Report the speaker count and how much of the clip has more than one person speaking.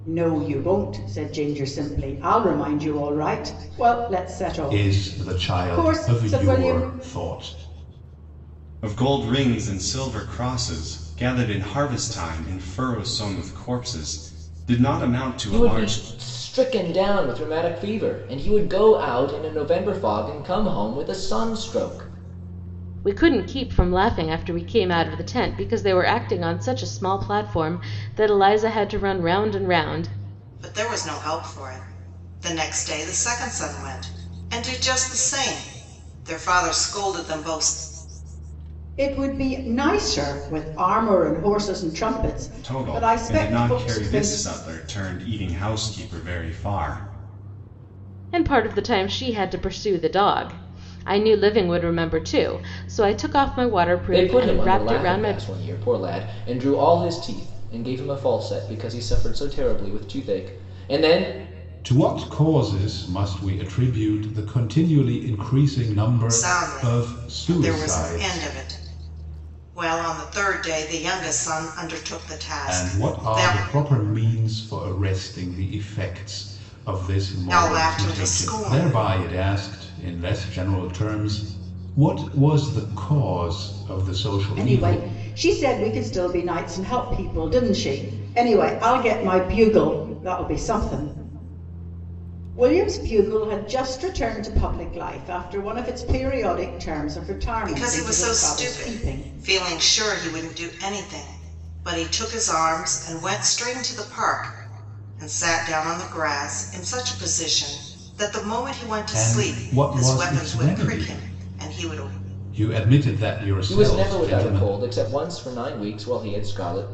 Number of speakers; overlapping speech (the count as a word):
six, about 14%